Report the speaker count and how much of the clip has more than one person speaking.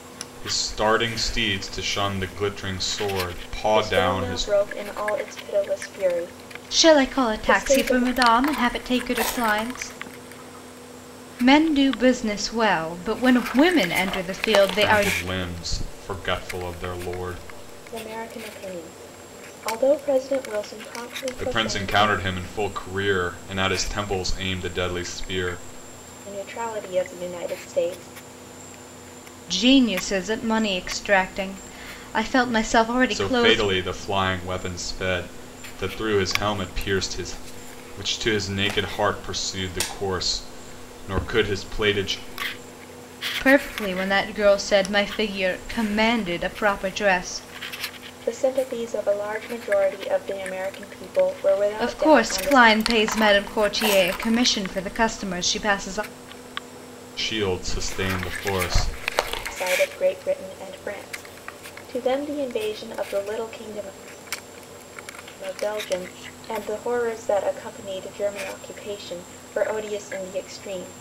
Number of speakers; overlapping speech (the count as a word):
three, about 7%